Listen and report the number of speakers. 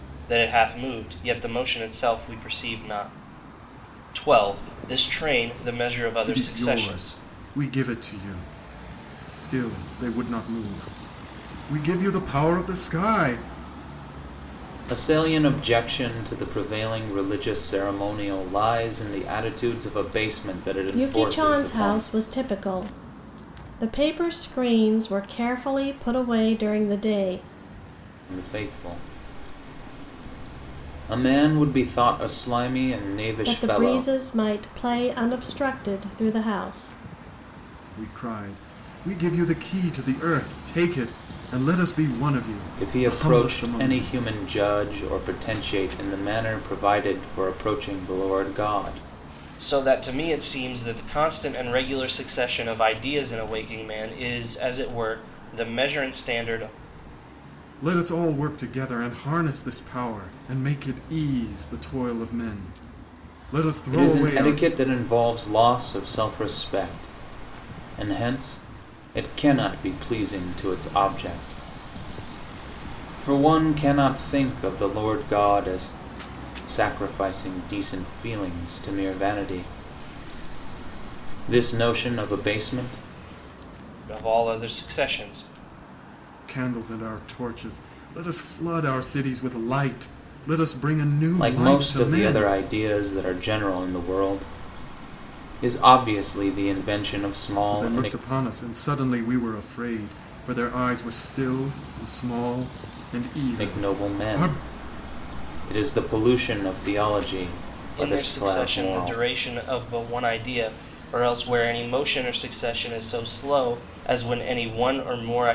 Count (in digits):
4